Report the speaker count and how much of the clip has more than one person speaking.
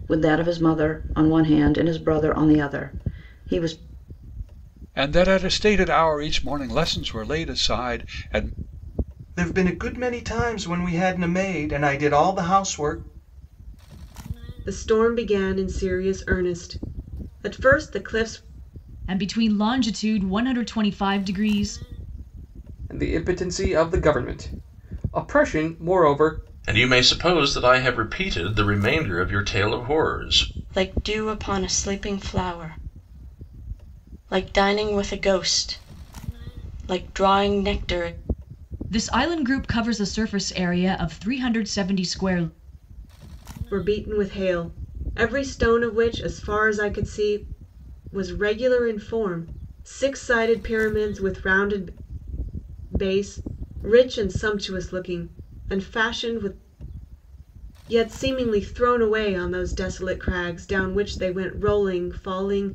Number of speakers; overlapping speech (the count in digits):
8, no overlap